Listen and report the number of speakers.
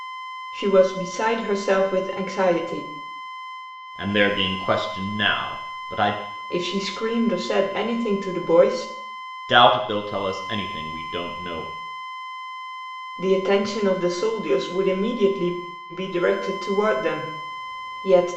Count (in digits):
2